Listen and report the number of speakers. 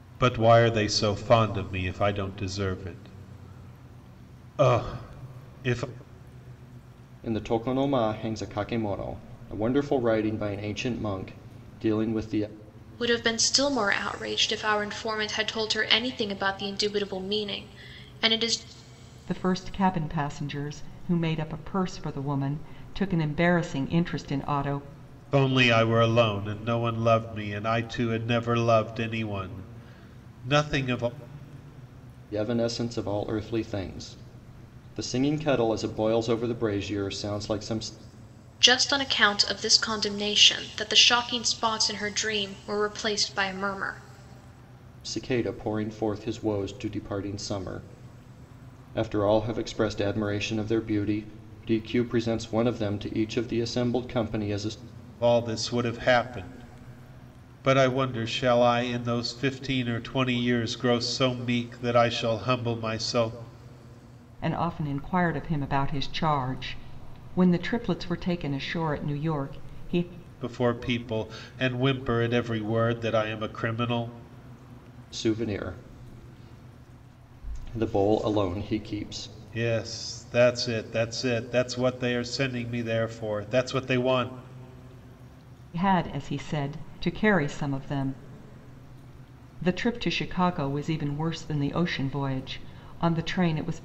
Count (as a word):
four